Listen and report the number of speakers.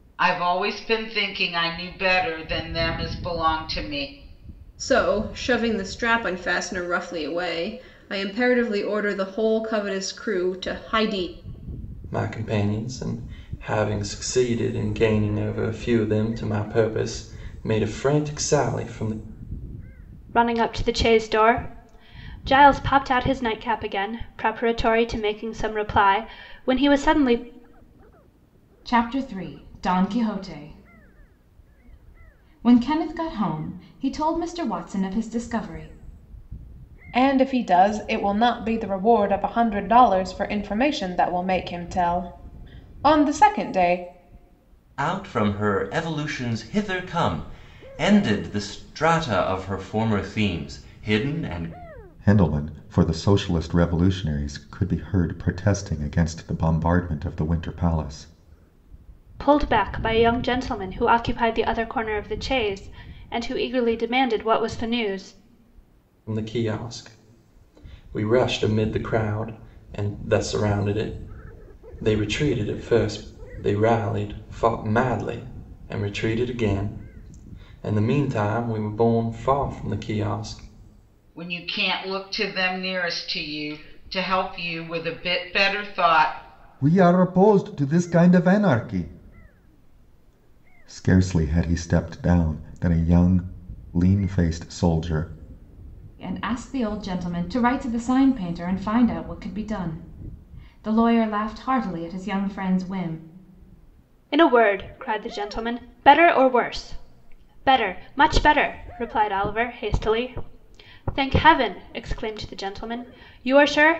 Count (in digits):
8